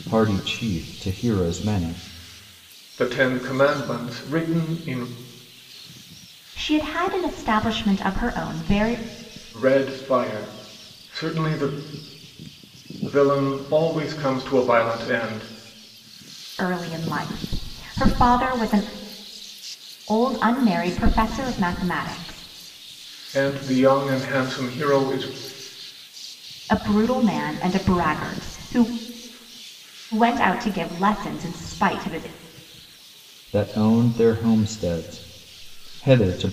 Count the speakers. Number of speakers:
3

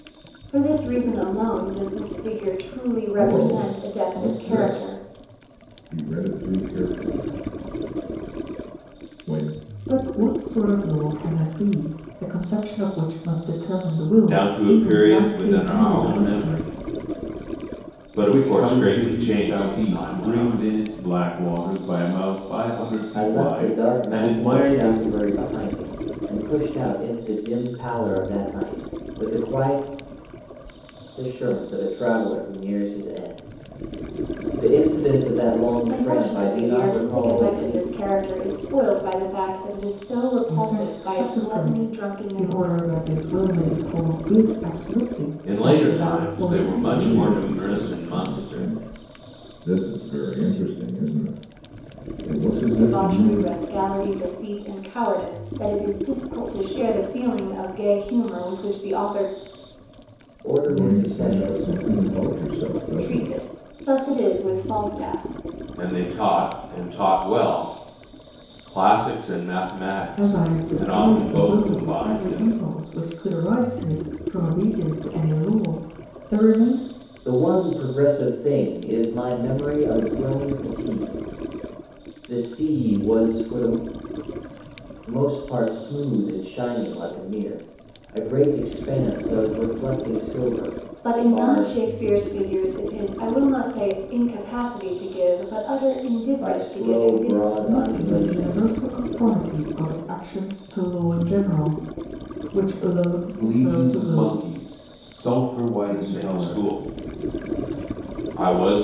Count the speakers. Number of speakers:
6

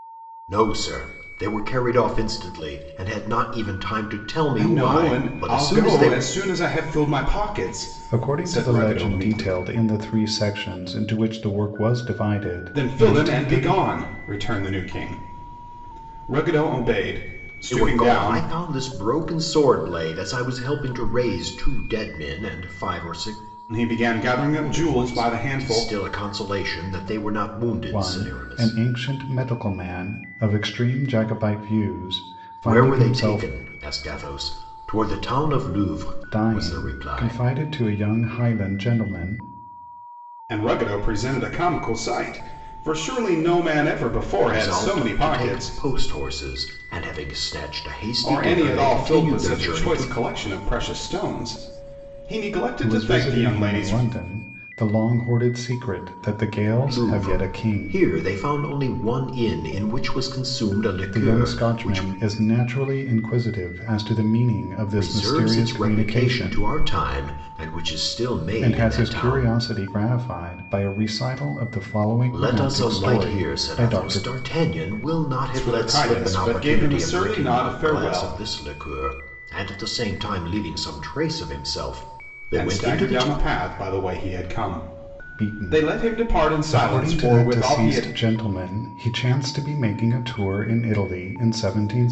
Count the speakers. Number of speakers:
3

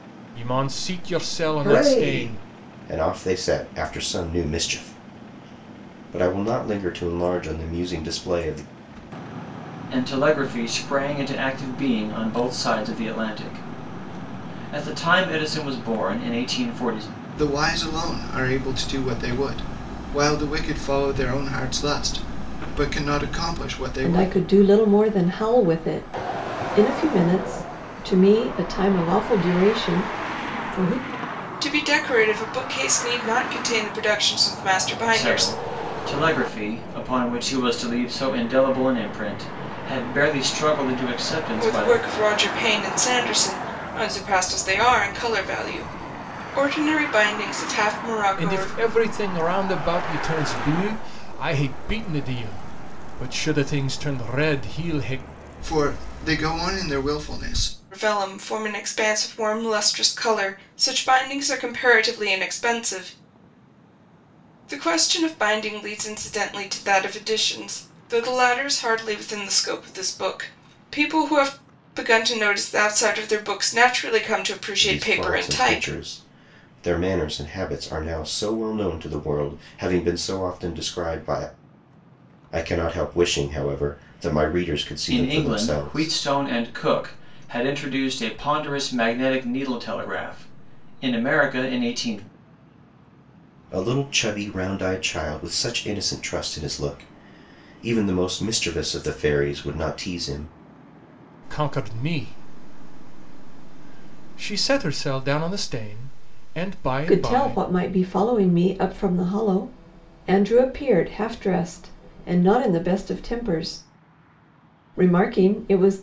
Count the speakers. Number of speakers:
6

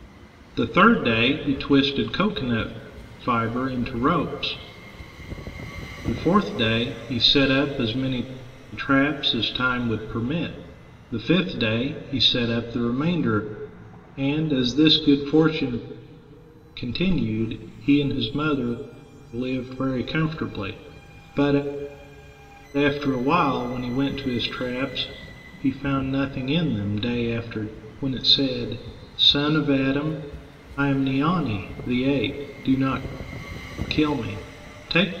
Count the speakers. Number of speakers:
1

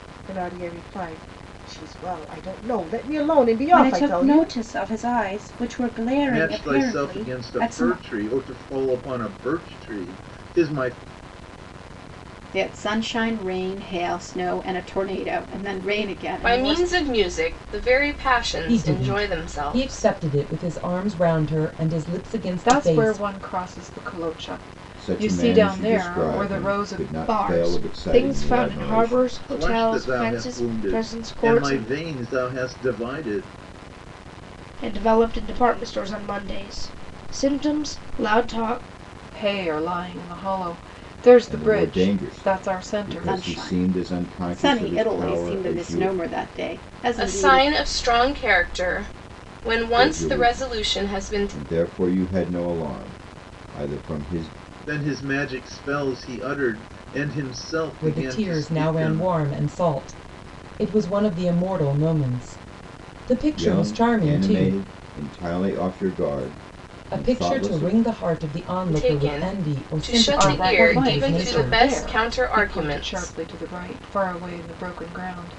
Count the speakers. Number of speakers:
9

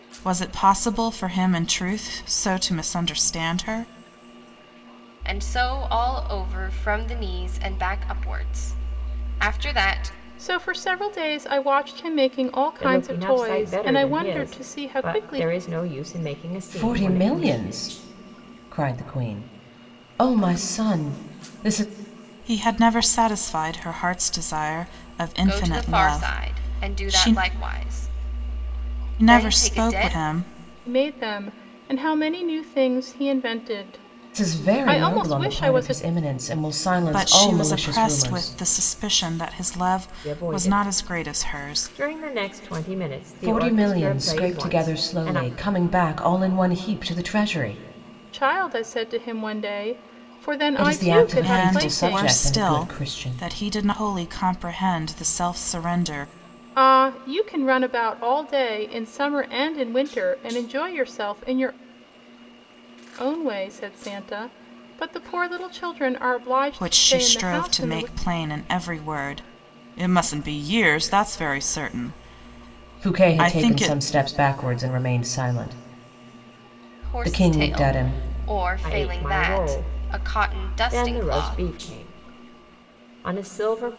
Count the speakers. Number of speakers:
5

